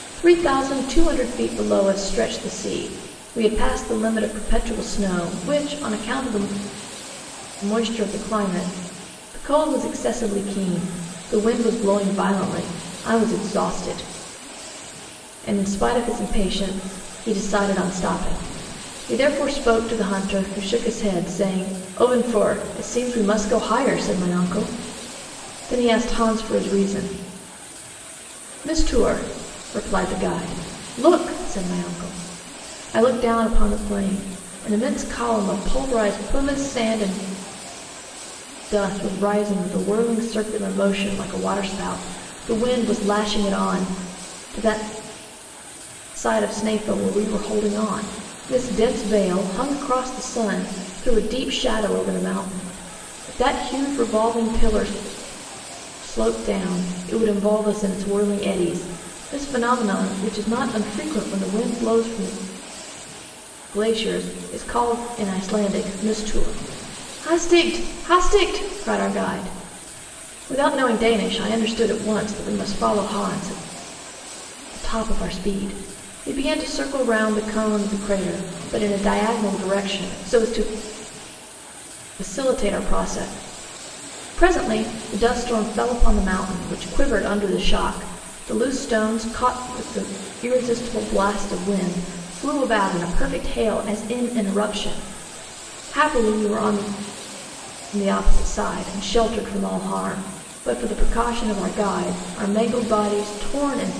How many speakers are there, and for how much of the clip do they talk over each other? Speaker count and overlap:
1, no overlap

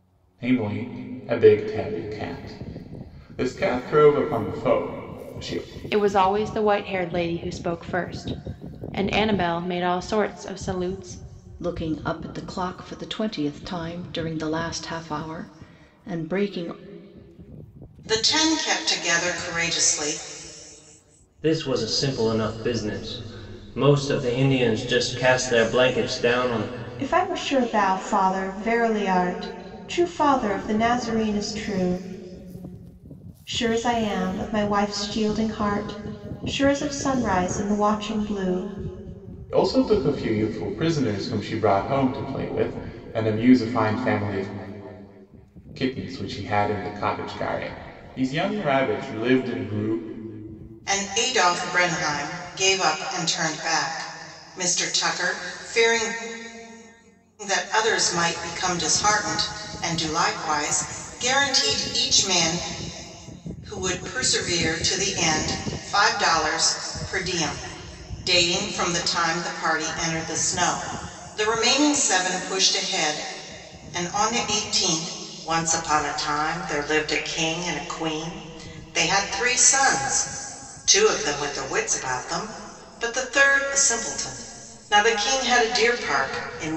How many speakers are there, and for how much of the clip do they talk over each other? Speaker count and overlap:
6, no overlap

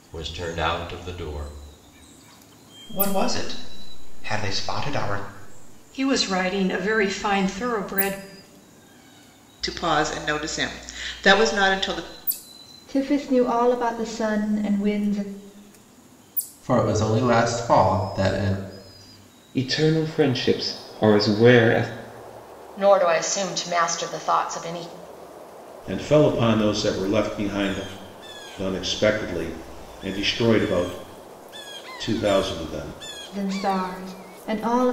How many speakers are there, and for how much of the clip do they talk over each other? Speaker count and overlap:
9, no overlap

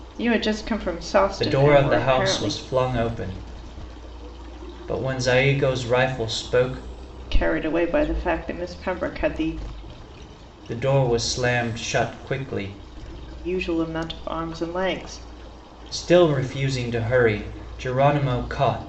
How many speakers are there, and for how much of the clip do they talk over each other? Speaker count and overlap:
2, about 7%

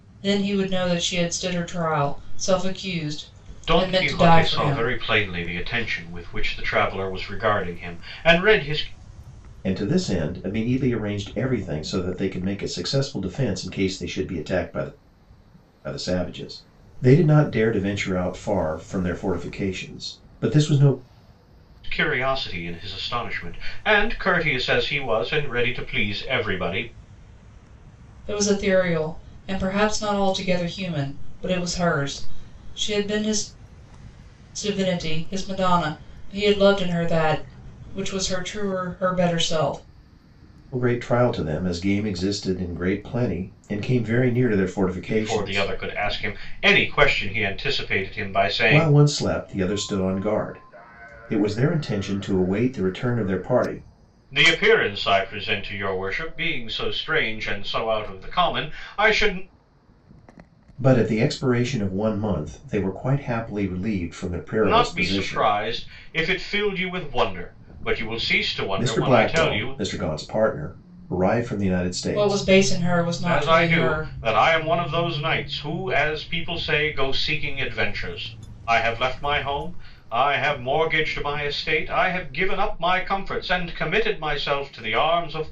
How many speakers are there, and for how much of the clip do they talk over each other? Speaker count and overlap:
3, about 6%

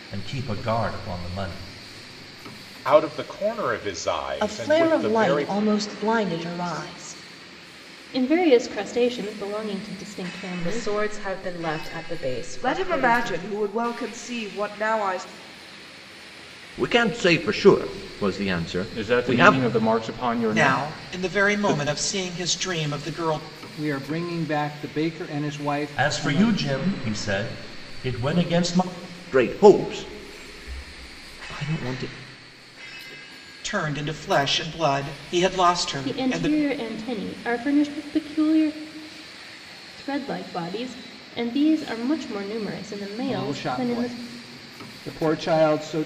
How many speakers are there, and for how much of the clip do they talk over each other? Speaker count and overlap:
10, about 14%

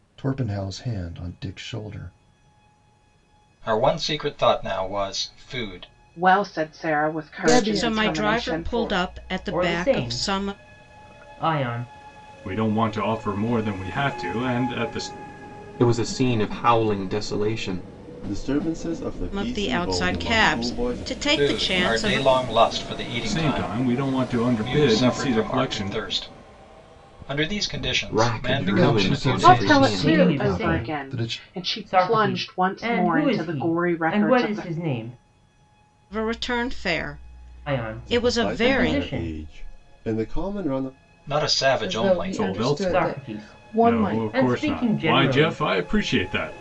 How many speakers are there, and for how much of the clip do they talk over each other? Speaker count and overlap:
9, about 41%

